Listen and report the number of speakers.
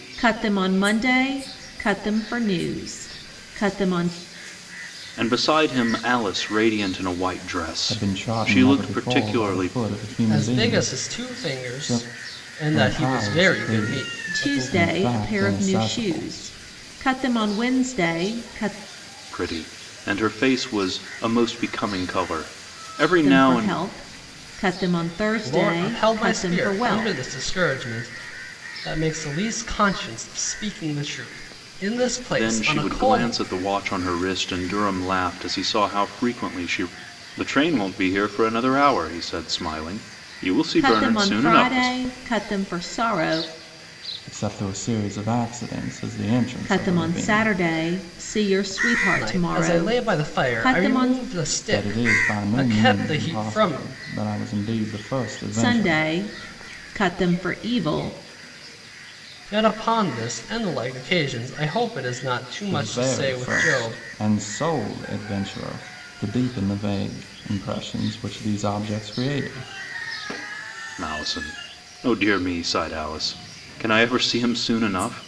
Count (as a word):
four